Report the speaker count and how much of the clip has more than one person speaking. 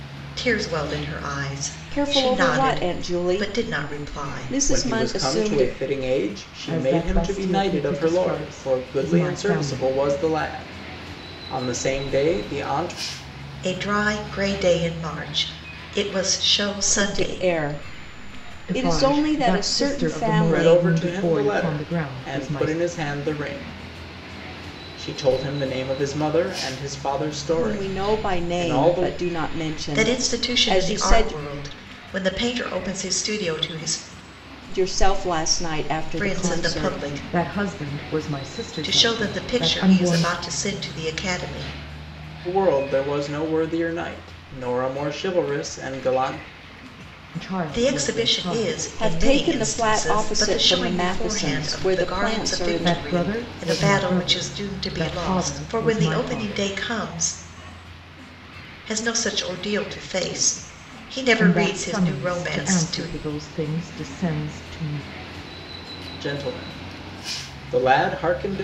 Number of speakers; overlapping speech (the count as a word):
four, about 42%